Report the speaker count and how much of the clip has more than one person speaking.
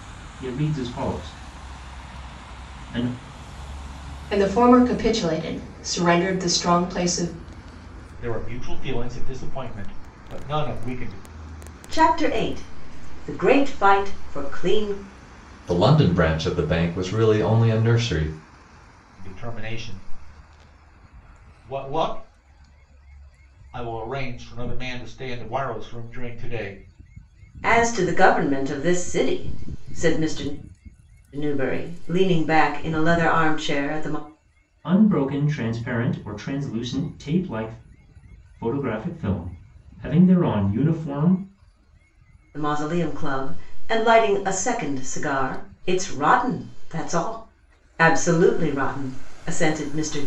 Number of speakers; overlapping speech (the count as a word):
five, no overlap